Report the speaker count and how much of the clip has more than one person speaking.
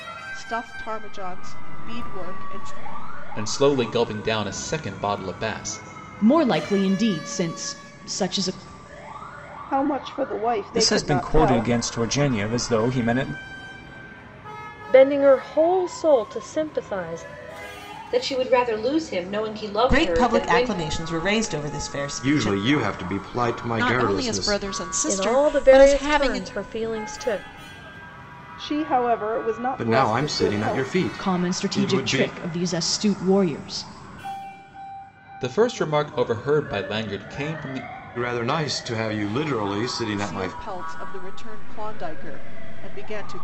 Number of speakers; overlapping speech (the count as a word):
ten, about 17%